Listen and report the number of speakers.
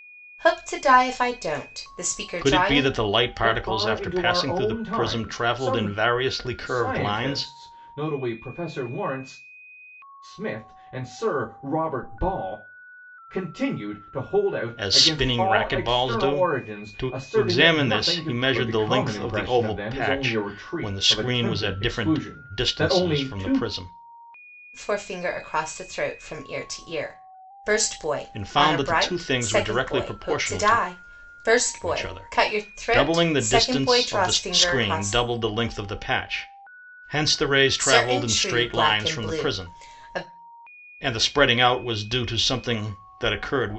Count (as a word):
three